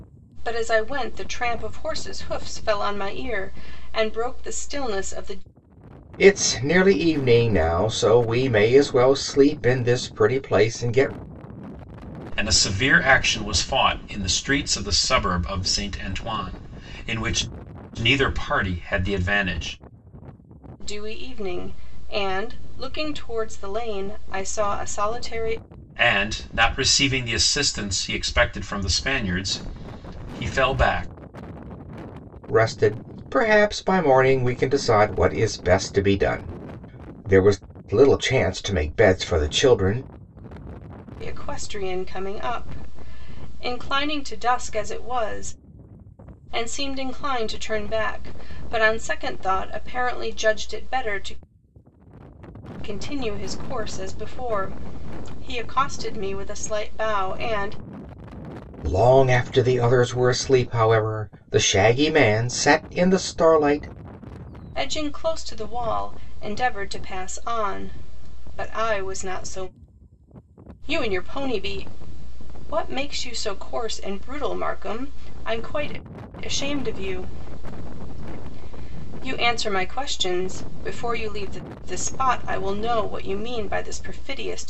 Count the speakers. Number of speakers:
three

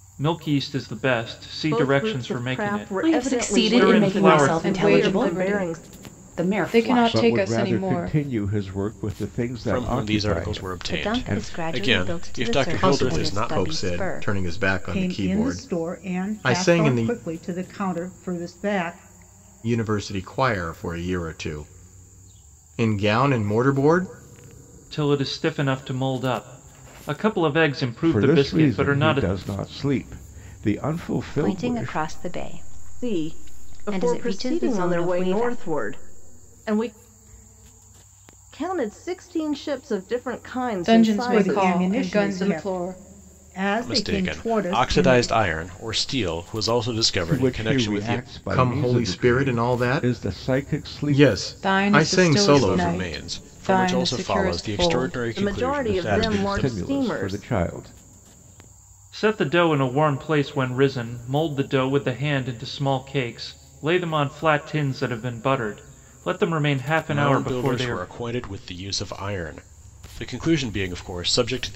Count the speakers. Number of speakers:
nine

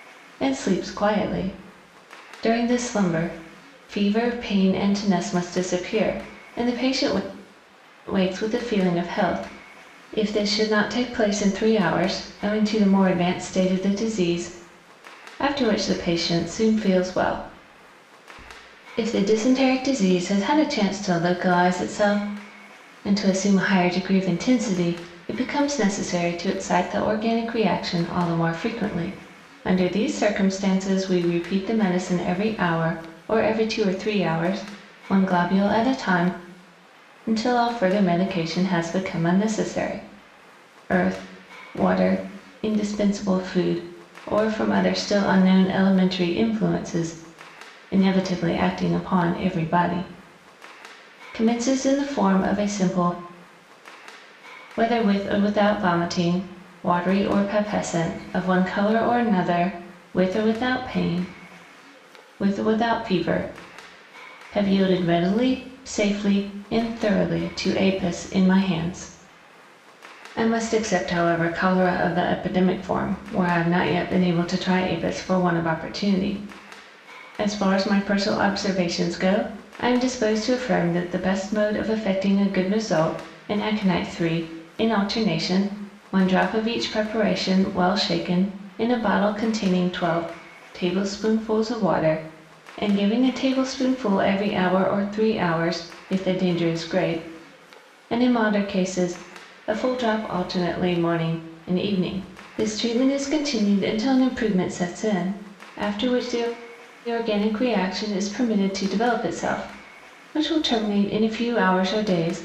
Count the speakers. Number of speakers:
one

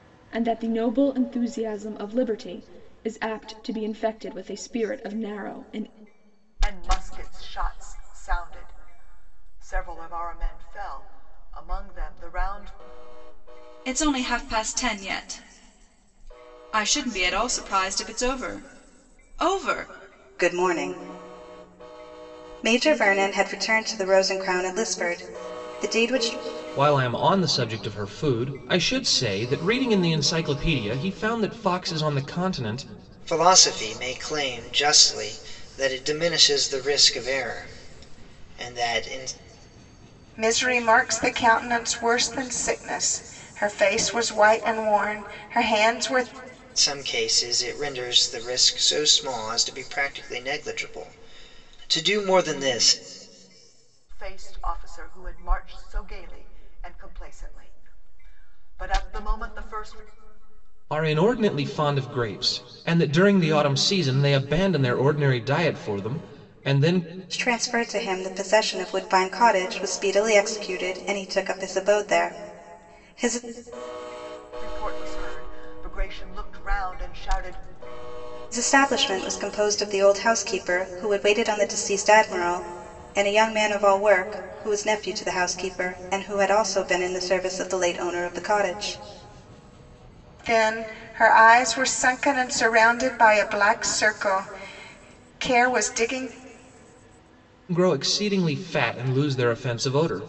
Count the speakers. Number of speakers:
seven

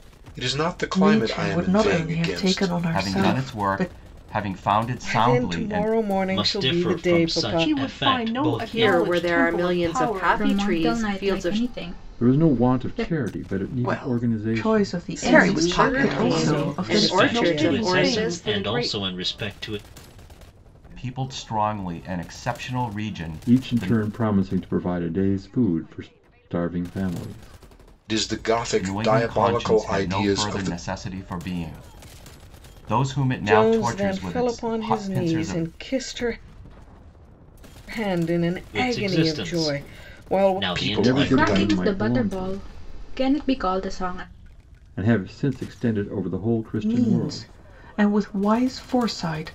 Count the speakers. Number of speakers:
ten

